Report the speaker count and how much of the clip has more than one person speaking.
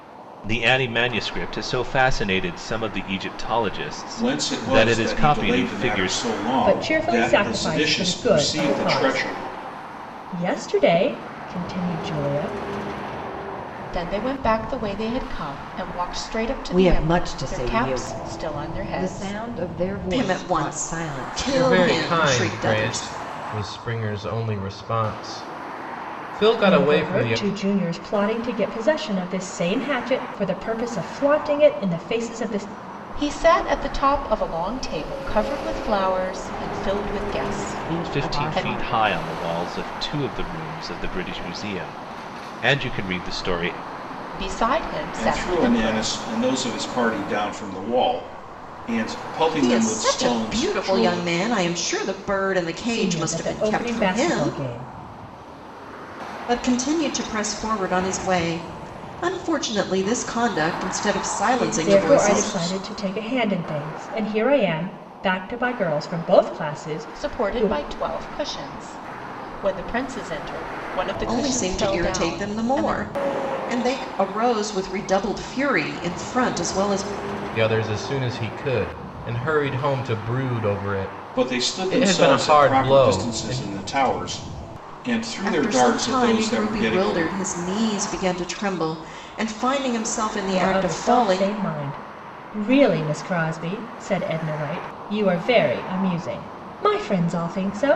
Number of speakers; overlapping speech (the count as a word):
seven, about 27%